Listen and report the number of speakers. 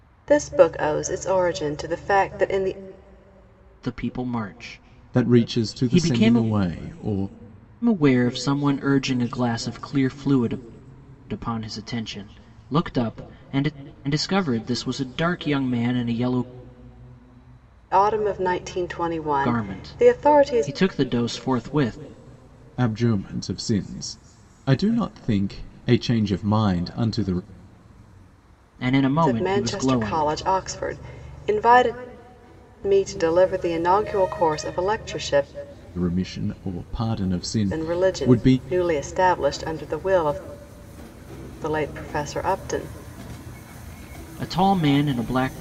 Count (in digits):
3